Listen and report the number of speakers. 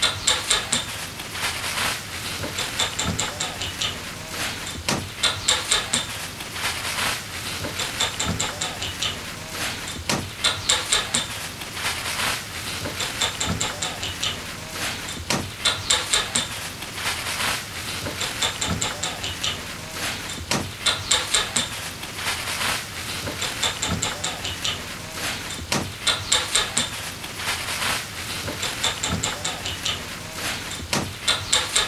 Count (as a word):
zero